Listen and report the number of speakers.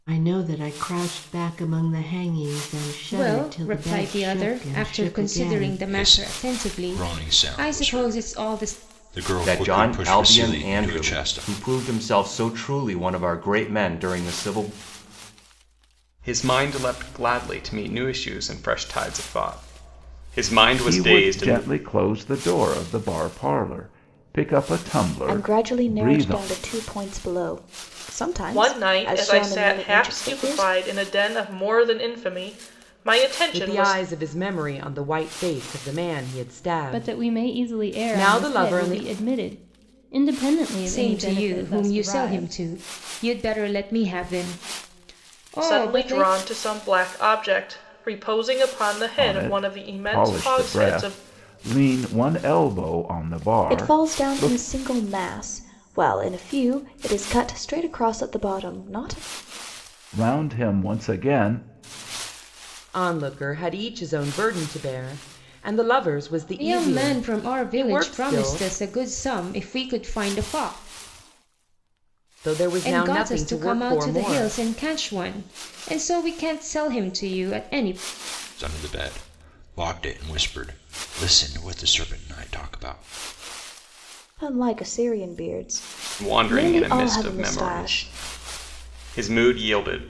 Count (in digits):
10